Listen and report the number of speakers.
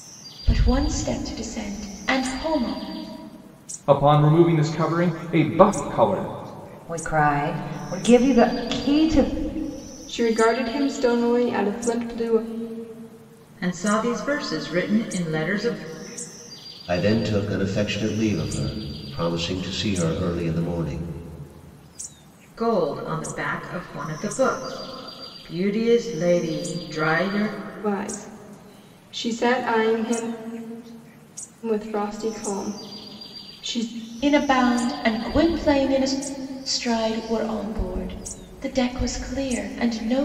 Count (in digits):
6